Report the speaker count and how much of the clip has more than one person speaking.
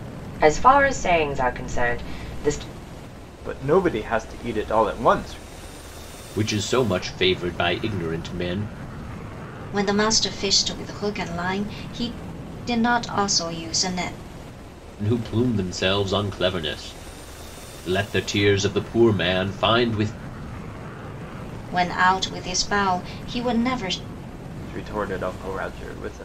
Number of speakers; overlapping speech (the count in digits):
4, no overlap